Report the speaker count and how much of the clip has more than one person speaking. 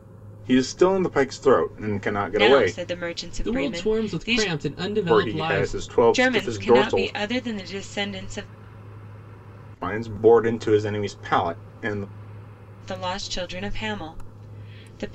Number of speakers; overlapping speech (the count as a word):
three, about 23%